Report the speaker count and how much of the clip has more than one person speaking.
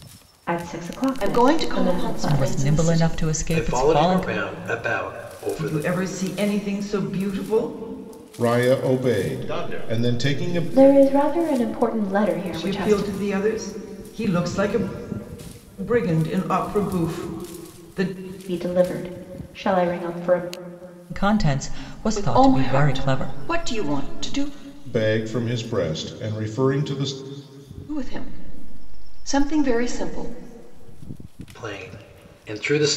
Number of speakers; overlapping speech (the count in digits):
7, about 22%